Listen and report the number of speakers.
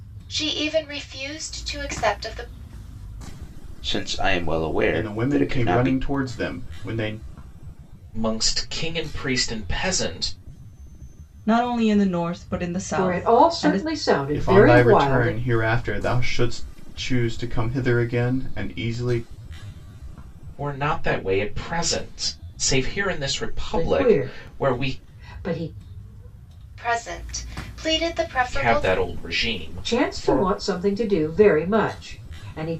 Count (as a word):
six